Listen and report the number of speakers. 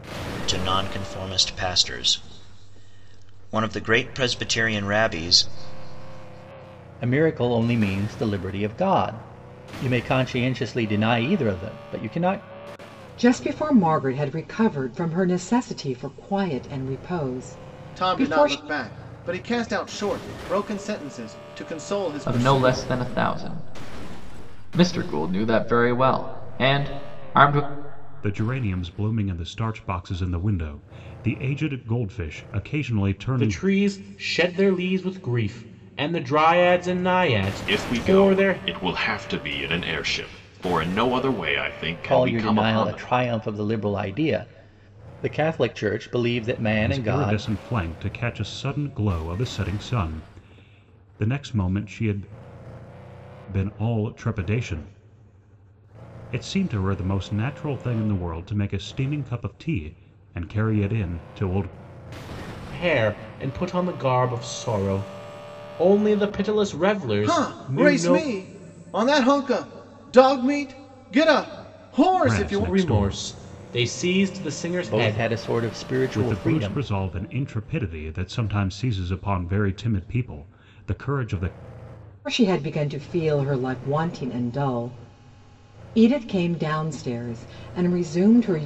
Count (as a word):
eight